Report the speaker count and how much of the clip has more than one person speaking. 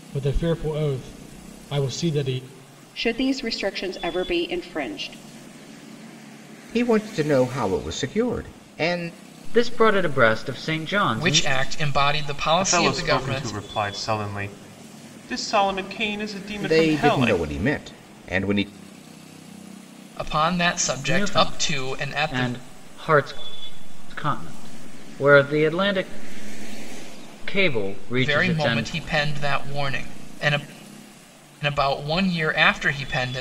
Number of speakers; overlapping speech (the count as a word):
six, about 14%